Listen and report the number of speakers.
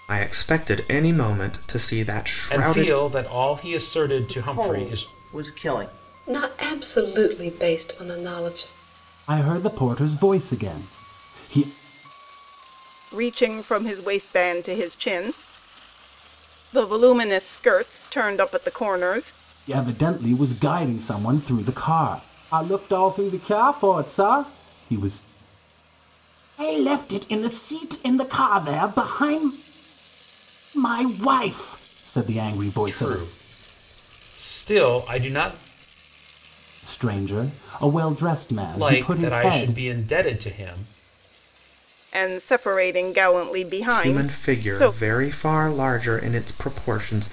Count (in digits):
6